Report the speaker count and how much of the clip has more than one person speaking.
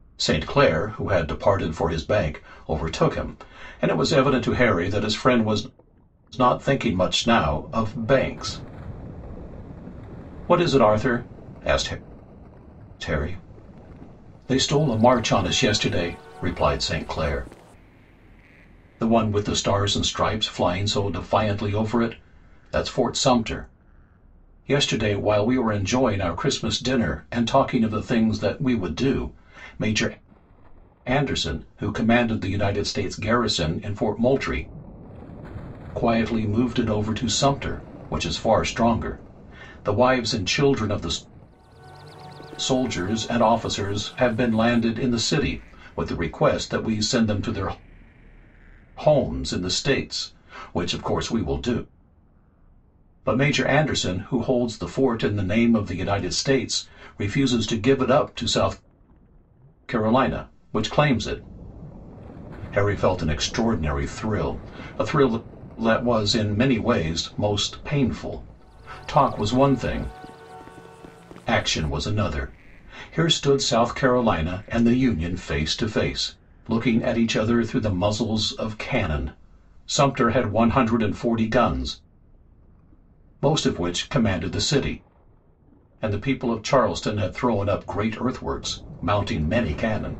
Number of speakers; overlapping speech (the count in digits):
1, no overlap